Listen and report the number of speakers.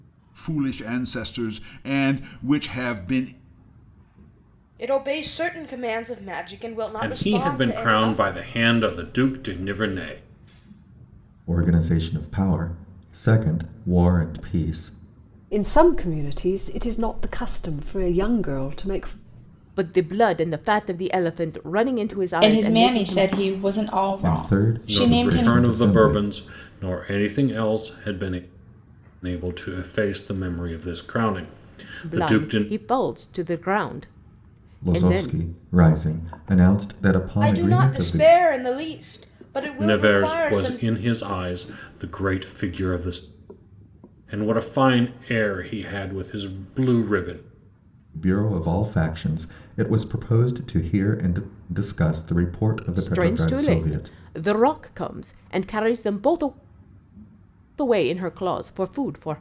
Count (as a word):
seven